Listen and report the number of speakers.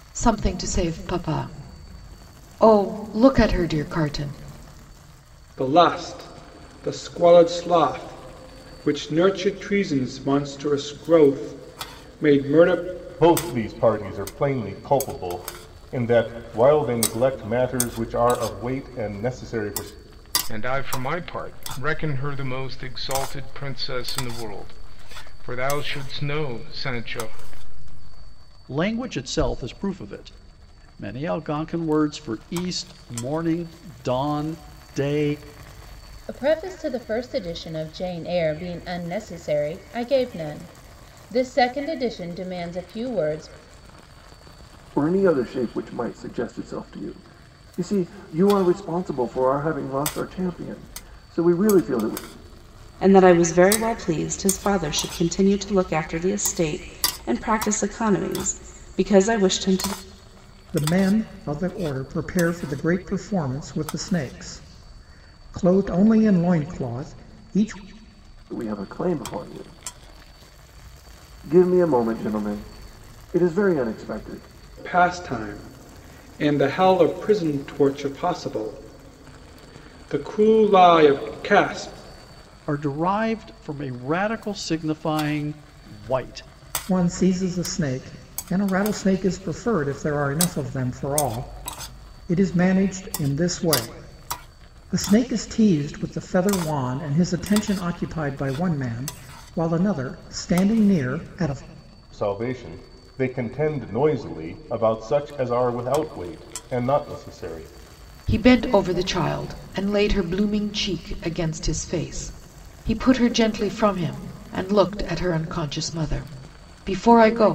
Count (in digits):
9